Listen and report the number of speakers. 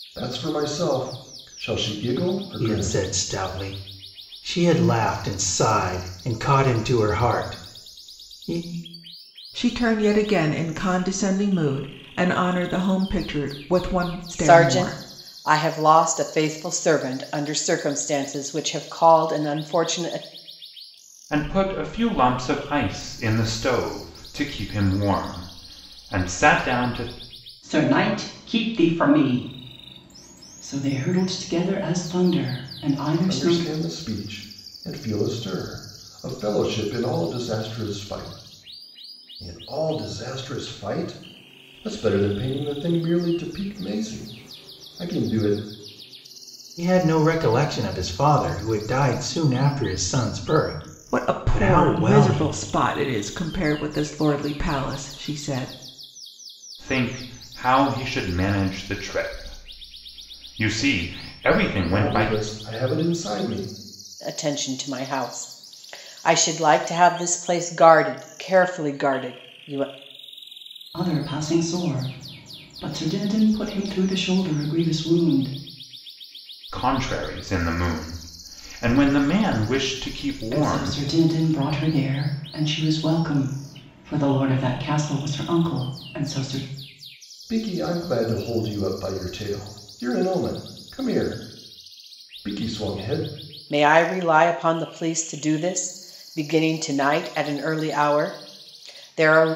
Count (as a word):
six